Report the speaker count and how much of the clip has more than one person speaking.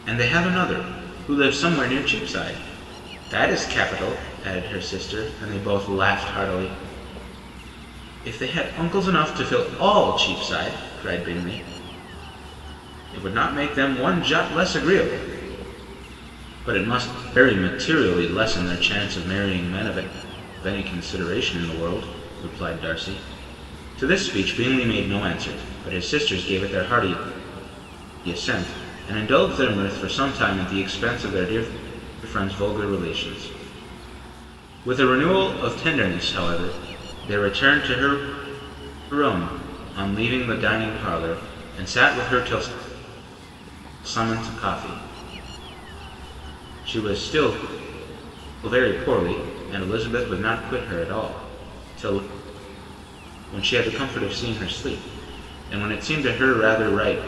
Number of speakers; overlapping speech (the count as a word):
one, no overlap